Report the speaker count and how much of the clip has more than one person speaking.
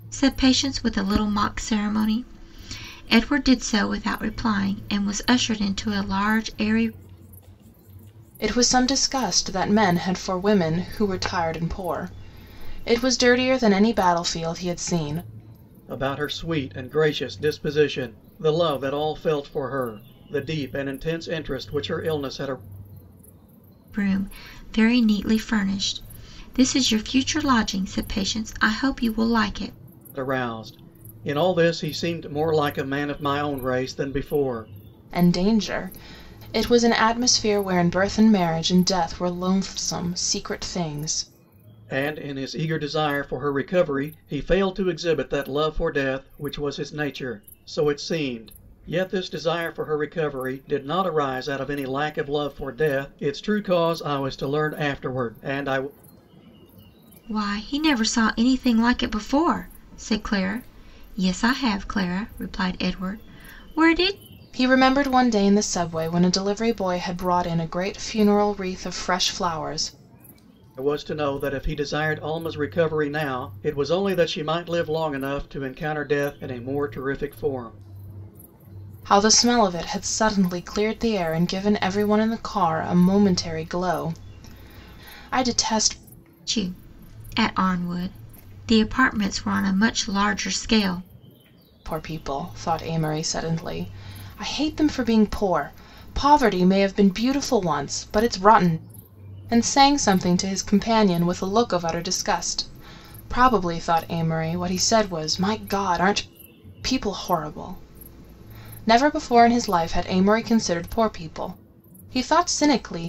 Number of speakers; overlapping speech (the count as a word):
three, no overlap